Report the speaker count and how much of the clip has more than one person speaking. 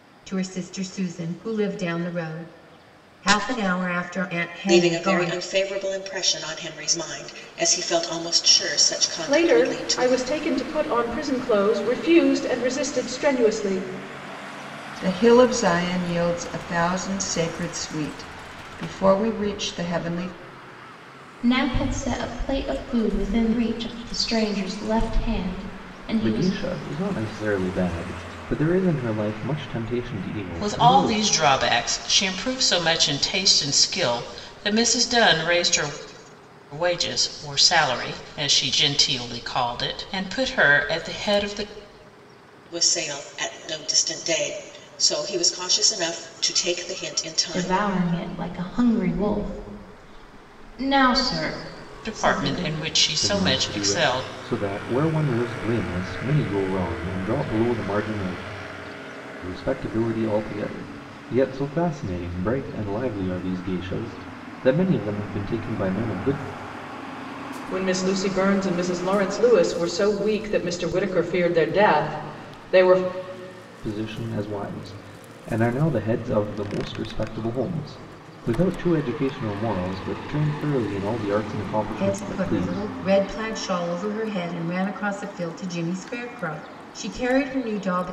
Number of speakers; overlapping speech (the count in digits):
7, about 7%